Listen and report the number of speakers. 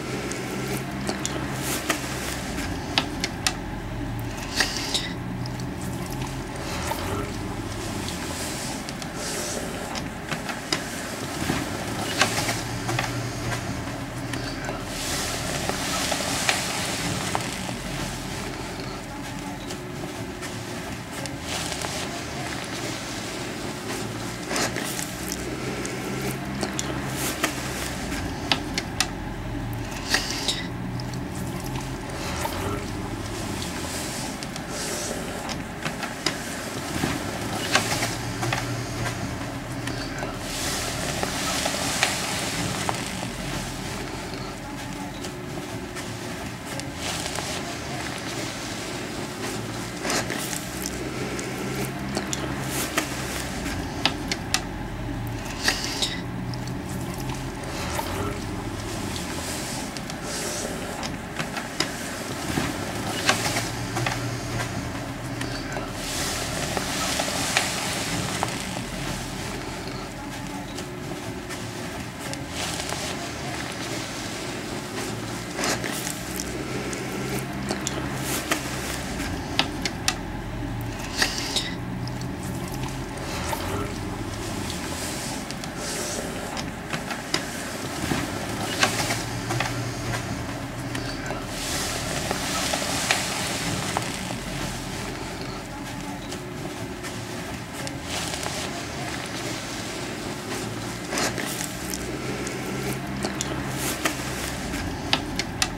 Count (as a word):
zero